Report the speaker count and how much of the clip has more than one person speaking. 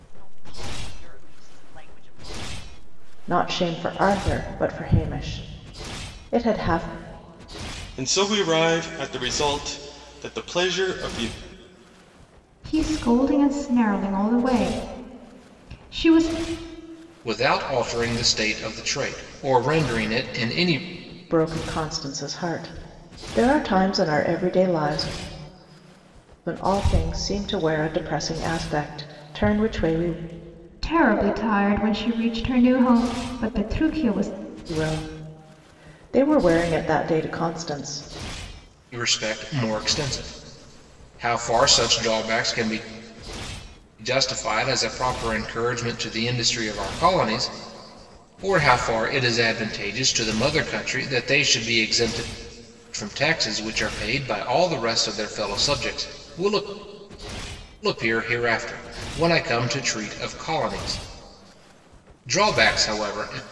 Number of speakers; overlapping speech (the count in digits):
5, no overlap